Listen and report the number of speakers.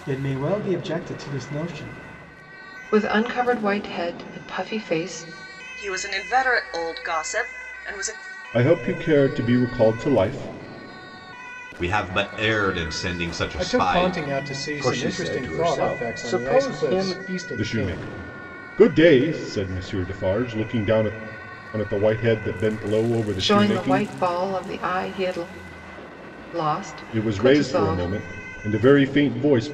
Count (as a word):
seven